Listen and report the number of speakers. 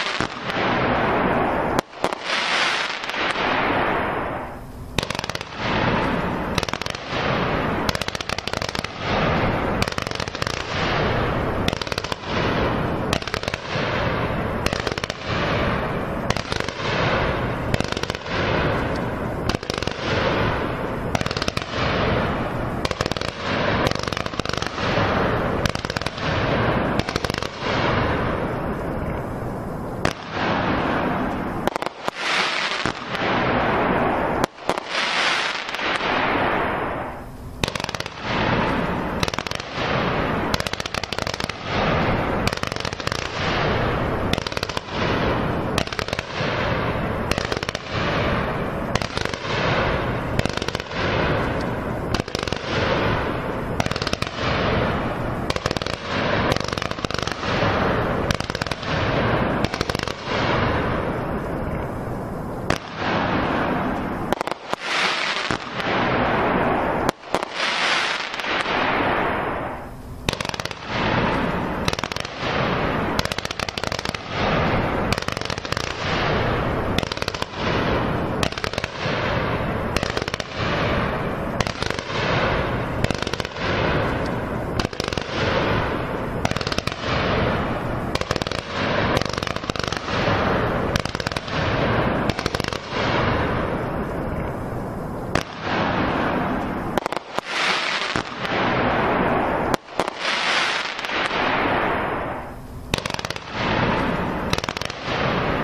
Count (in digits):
0